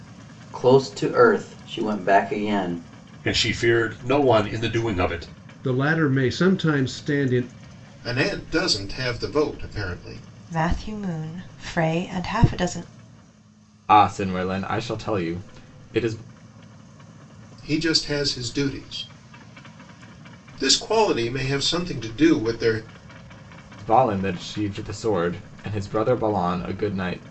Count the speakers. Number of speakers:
six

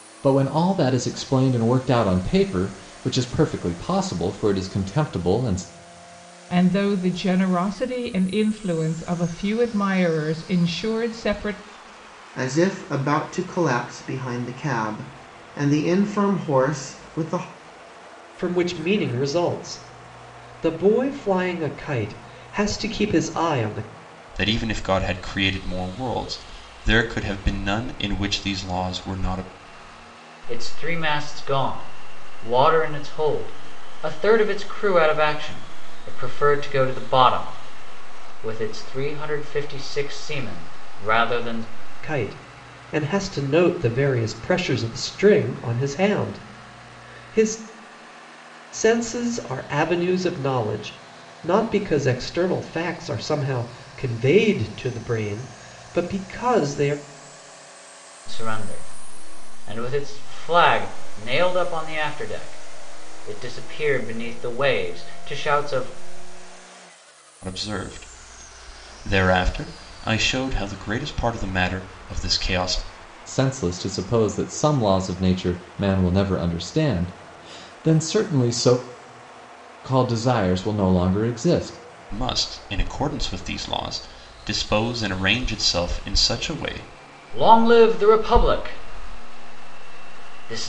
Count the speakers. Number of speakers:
six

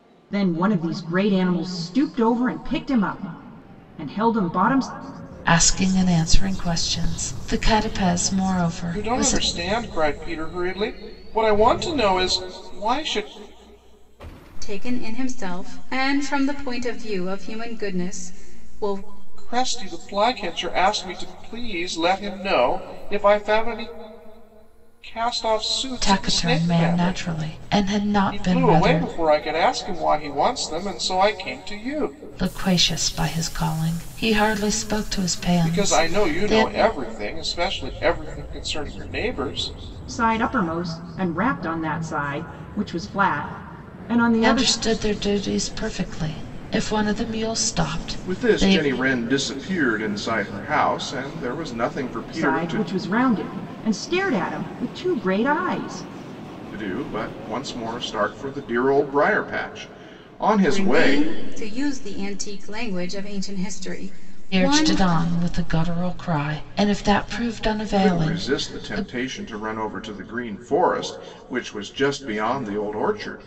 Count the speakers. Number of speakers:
four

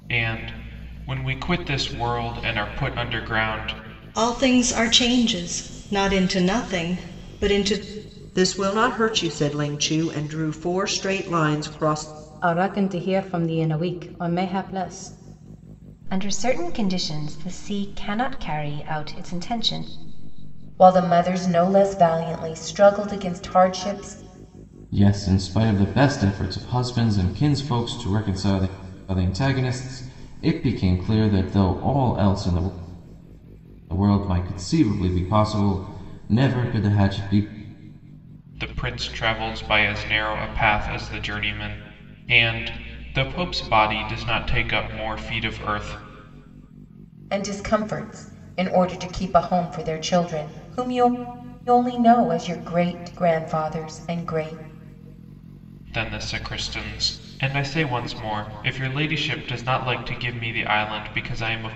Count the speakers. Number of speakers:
seven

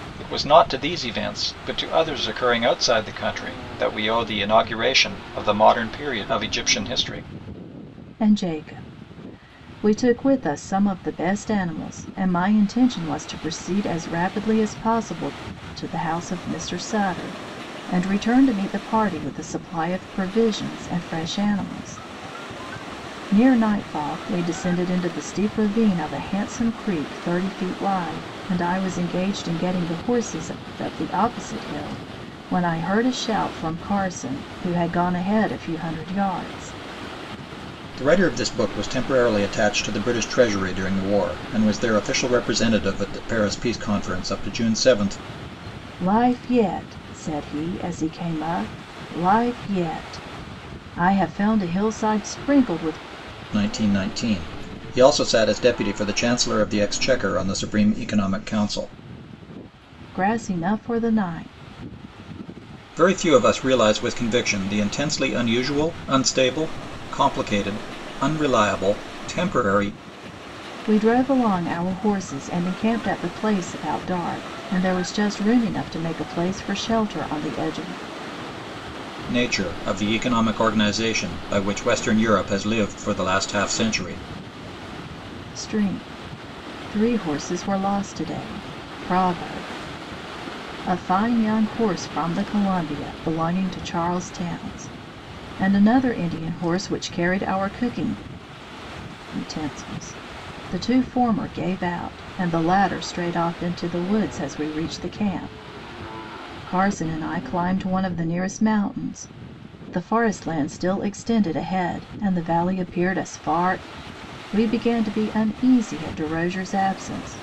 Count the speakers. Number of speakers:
two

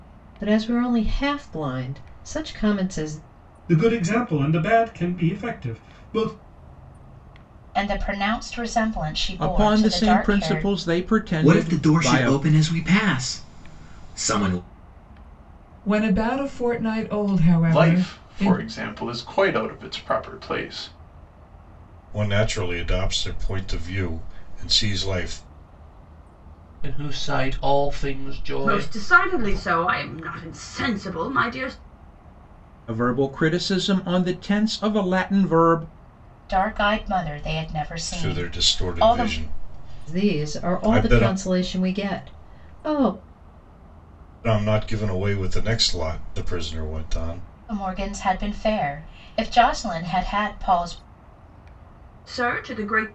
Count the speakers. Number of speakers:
ten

